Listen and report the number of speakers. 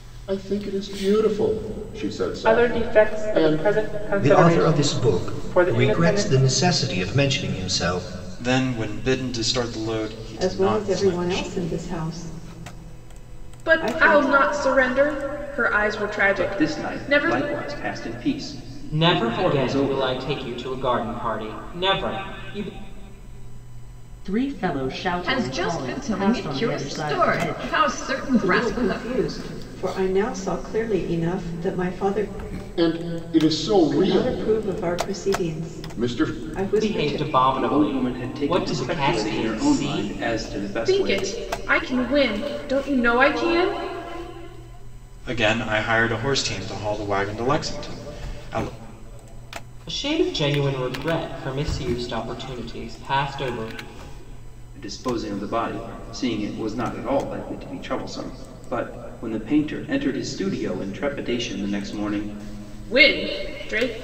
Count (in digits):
10